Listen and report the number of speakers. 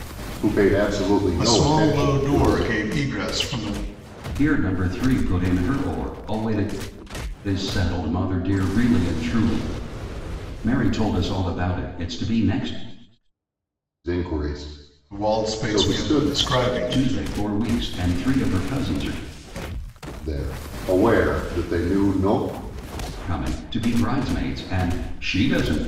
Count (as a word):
three